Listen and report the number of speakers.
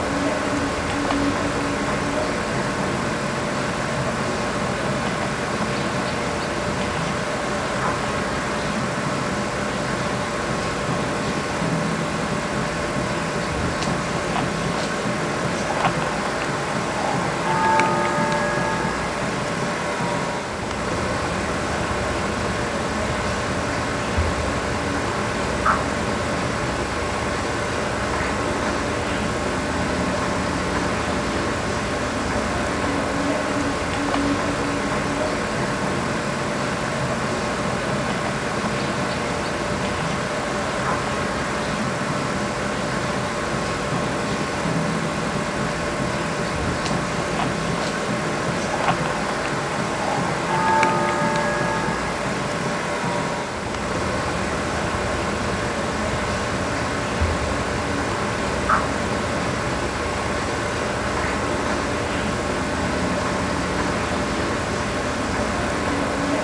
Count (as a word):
zero